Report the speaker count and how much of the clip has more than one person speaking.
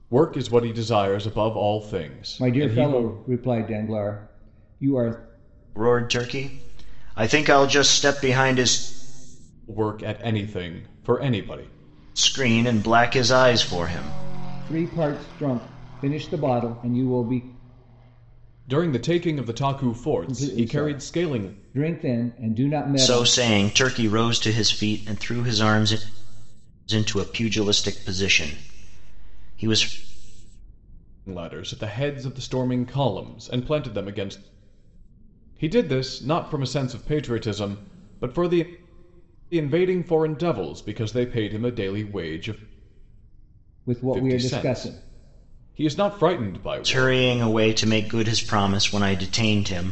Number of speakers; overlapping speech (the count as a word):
three, about 8%